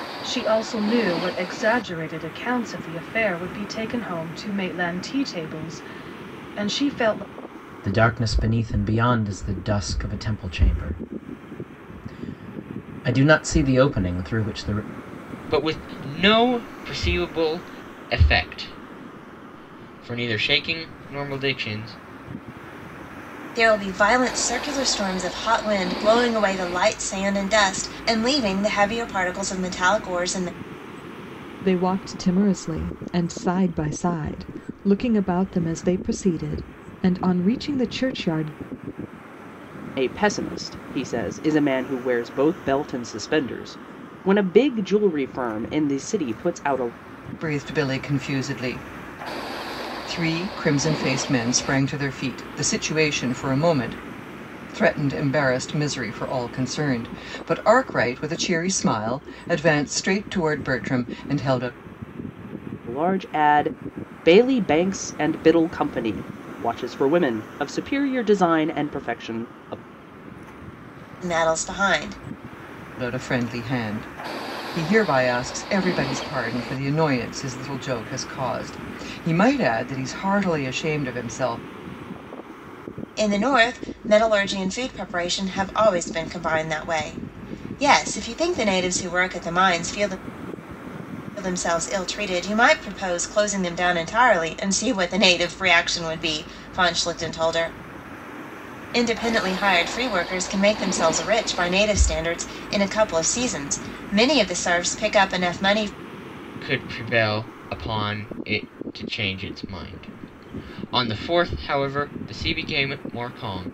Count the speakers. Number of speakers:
7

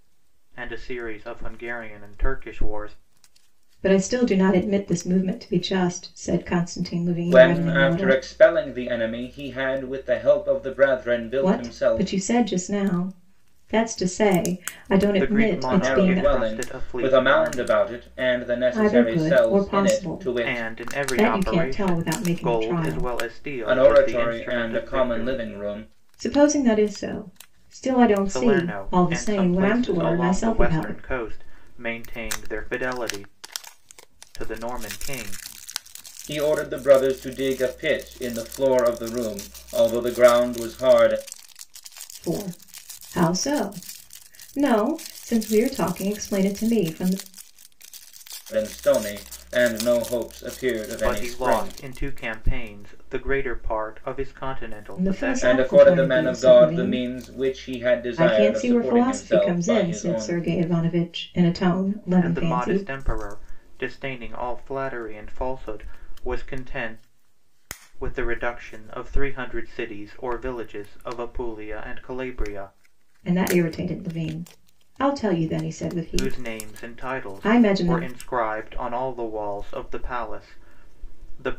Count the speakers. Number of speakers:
3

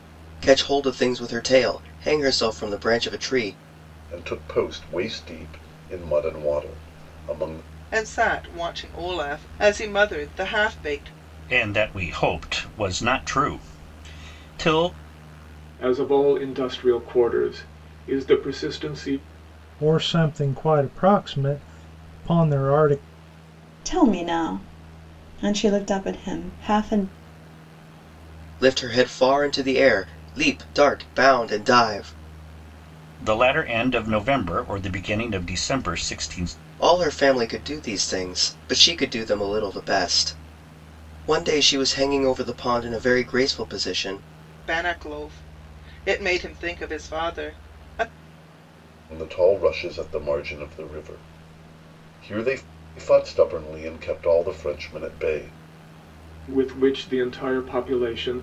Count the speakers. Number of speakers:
7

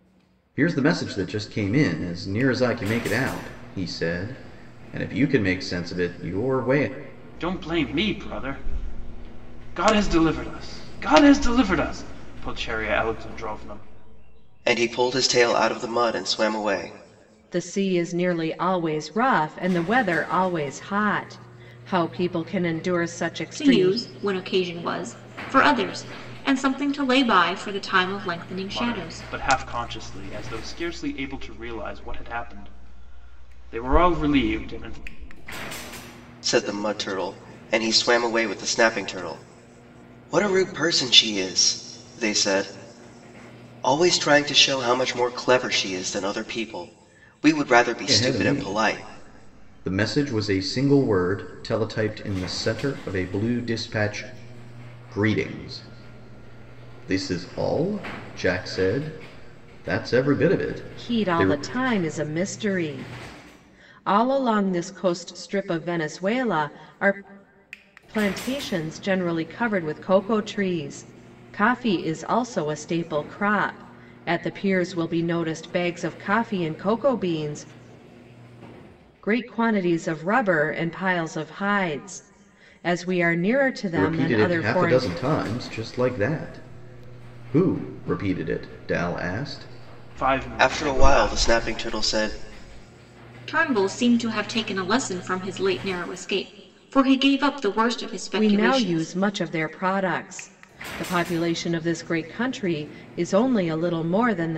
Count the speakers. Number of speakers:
5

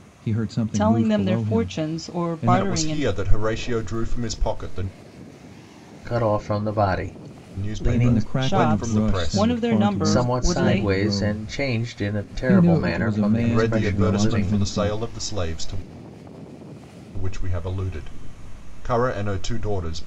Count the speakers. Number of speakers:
4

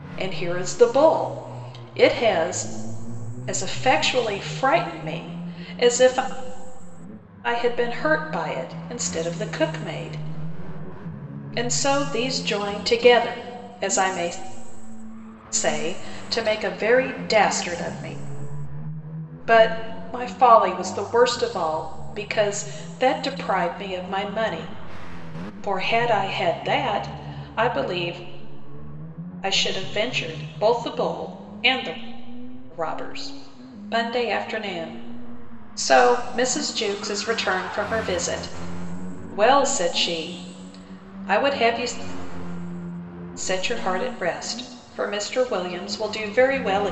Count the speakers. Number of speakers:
1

